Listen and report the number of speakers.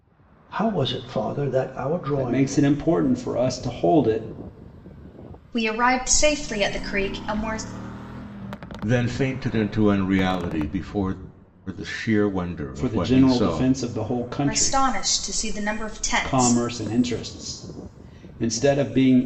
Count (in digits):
4